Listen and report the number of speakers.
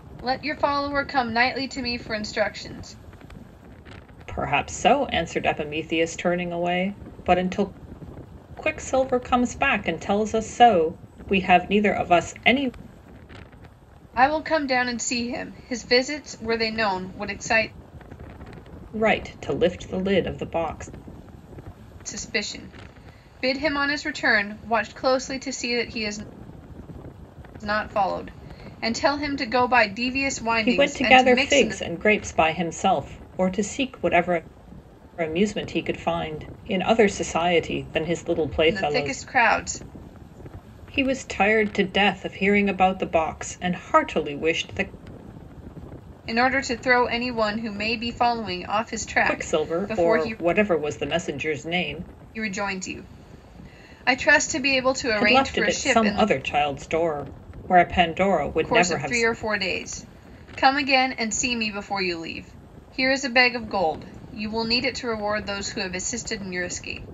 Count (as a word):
two